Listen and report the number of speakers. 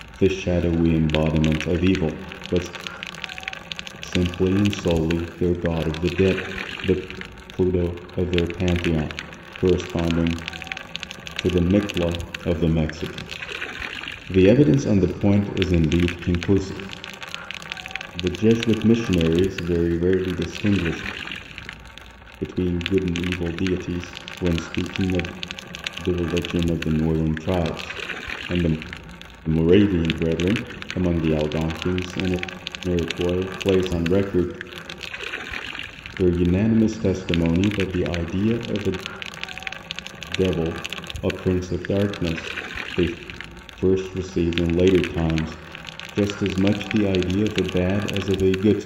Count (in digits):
1